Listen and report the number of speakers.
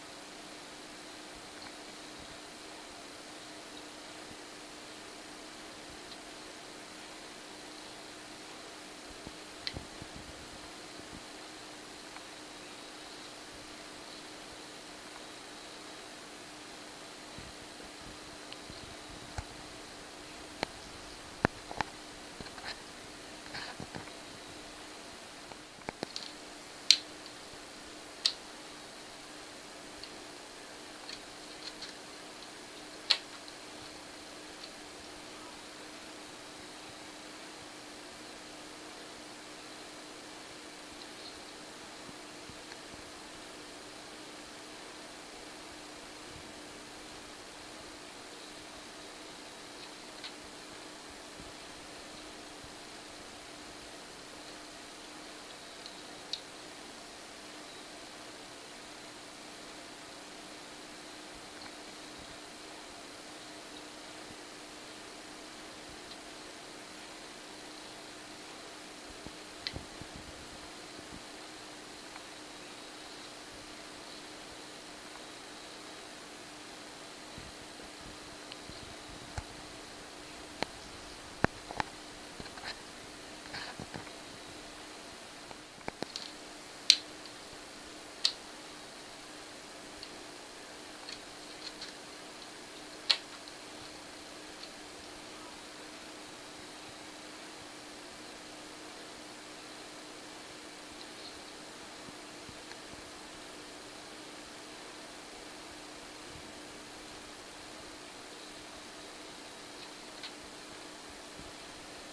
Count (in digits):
0